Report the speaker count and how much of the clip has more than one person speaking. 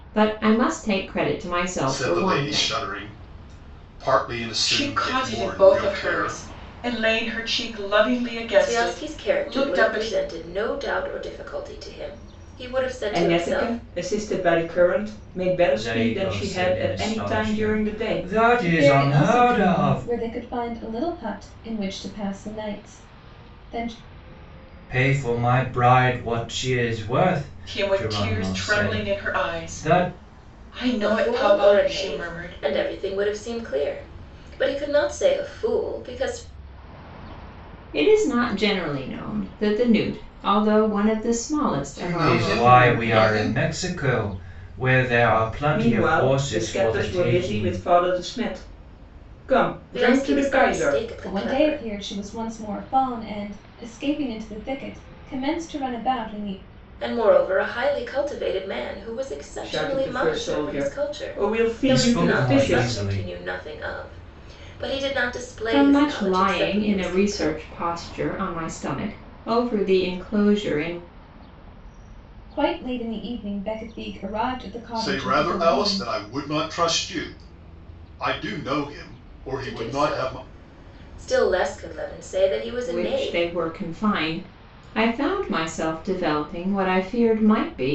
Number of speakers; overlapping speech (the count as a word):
seven, about 31%